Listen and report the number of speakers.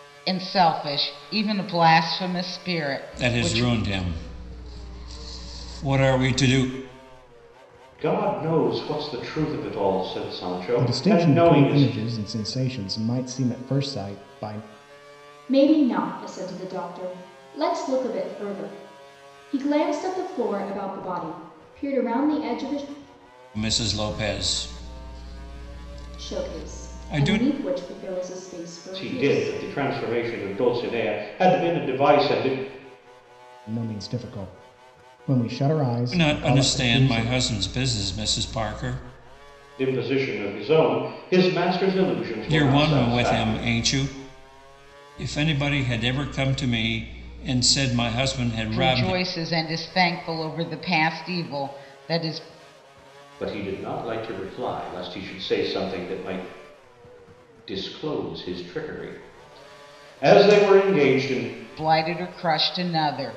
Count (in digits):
5